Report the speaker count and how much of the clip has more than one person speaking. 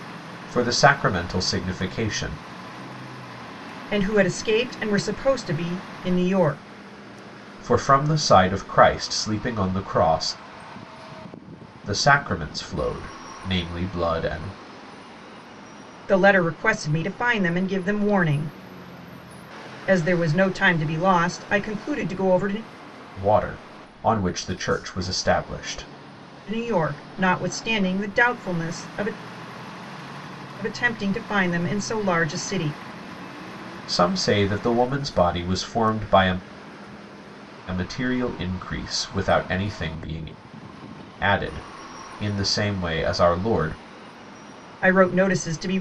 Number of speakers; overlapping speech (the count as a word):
two, no overlap